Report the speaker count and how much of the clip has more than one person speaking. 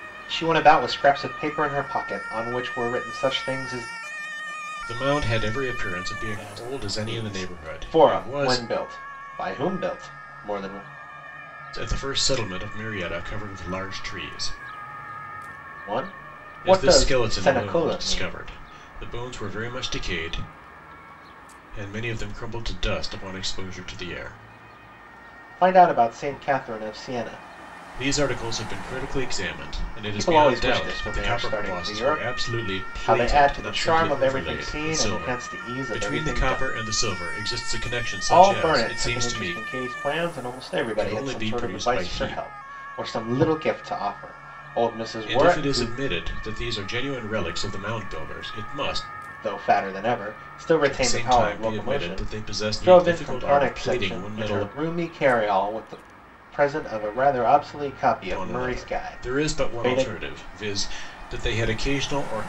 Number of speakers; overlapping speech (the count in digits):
2, about 29%